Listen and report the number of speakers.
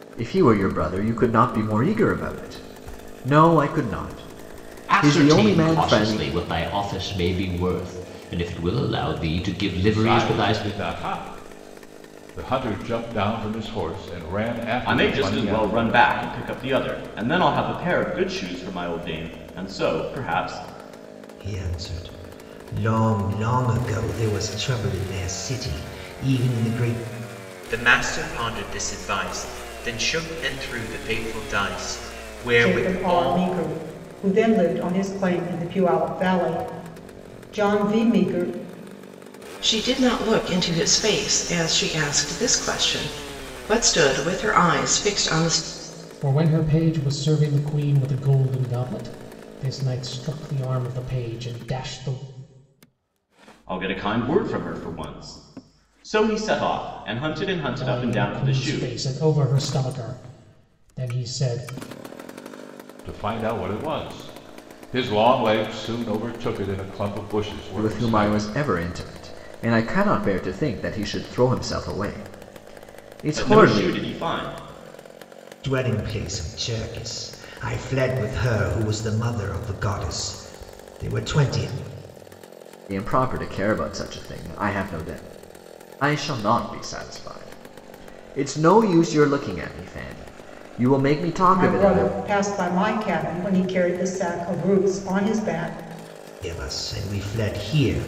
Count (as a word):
nine